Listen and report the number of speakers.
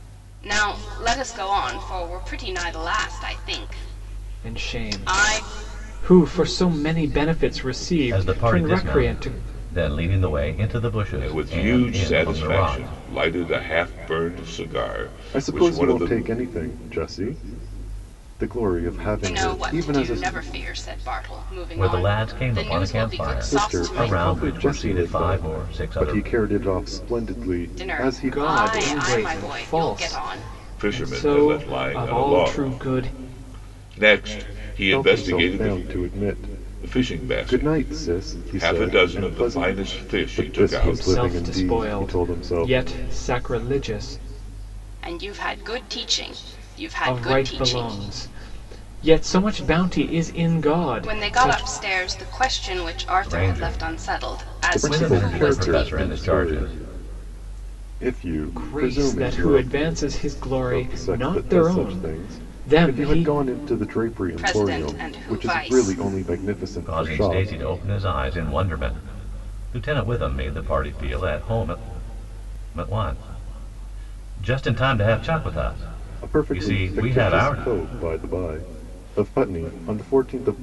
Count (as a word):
five